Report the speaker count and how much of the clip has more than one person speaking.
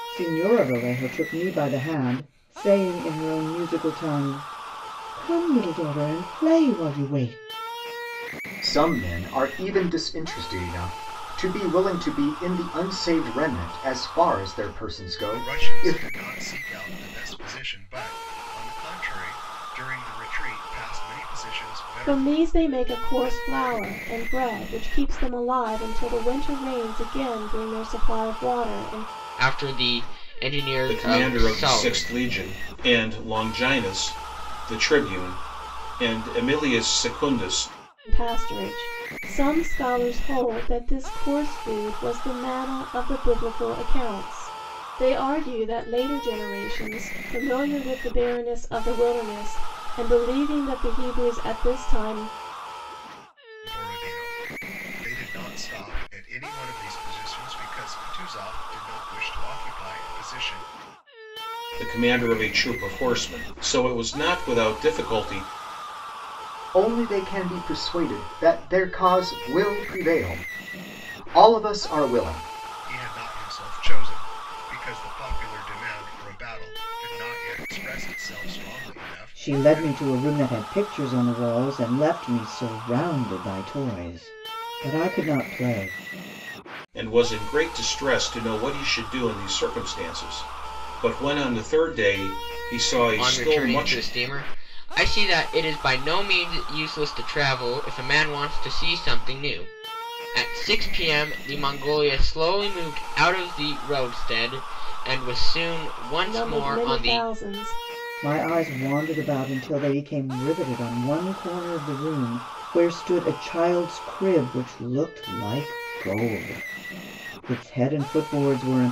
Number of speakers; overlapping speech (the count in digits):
6, about 4%